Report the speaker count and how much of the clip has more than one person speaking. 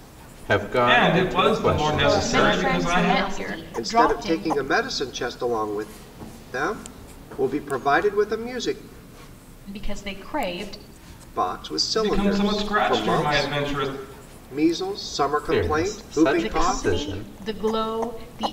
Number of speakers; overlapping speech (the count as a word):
five, about 38%